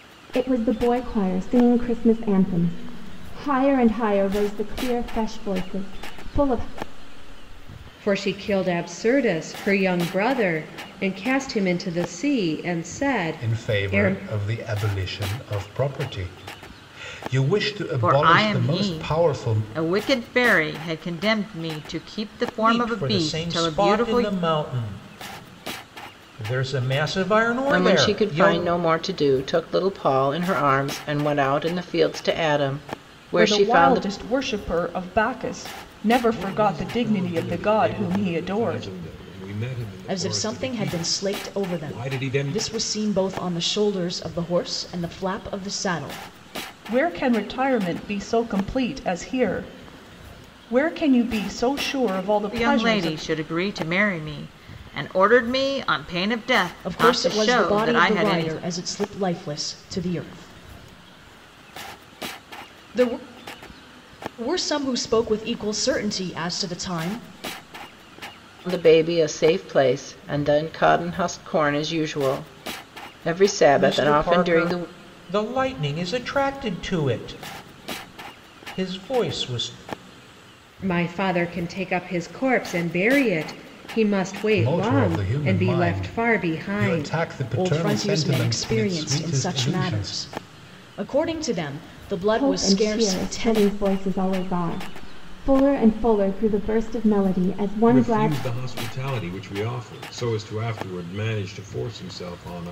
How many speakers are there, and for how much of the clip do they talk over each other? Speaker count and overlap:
9, about 21%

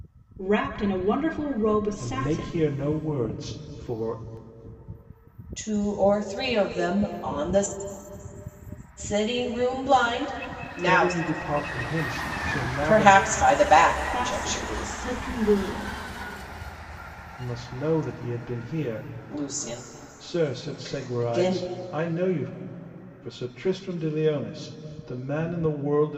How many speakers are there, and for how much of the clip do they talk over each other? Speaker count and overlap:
3, about 14%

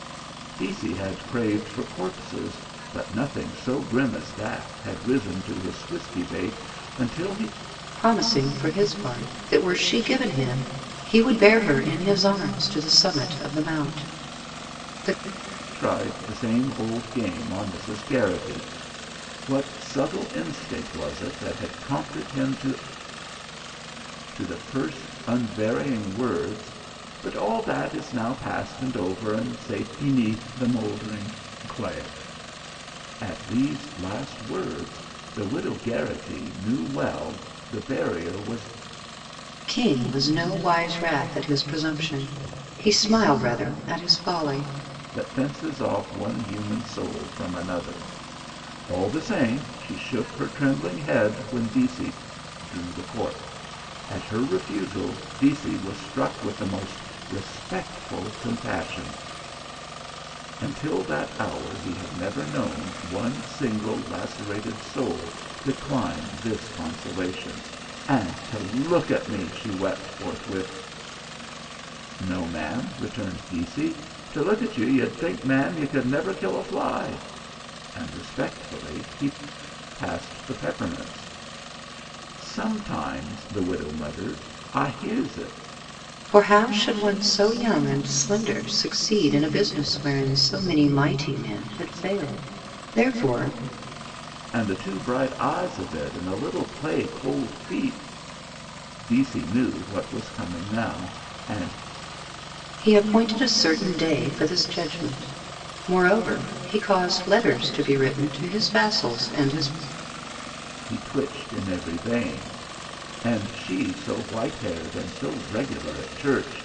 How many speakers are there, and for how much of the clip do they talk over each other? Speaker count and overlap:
2, no overlap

